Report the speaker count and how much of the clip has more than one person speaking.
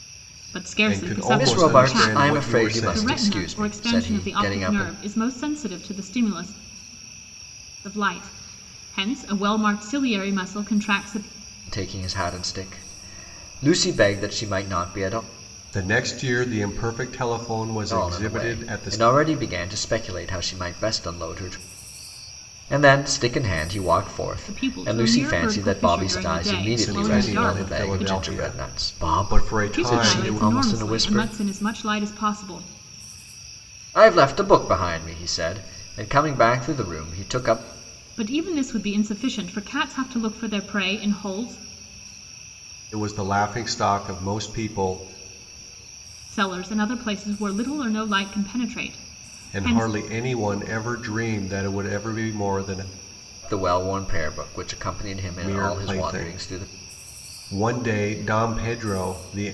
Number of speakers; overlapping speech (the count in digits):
3, about 24%